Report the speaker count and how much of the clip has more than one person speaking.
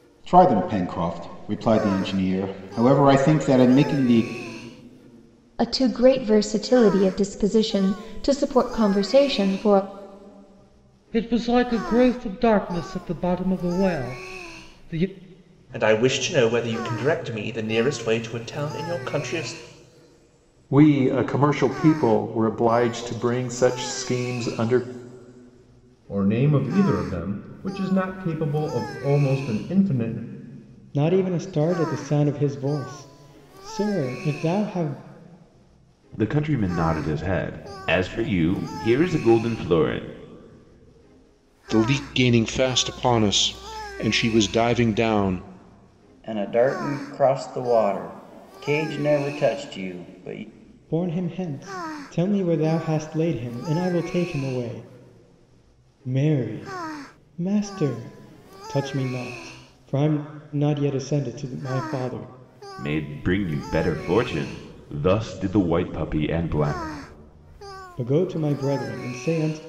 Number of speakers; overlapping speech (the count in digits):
10, no overlap